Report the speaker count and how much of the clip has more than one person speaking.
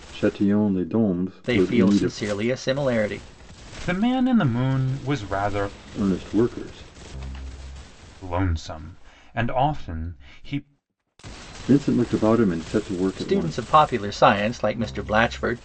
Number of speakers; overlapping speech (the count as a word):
three, about 9%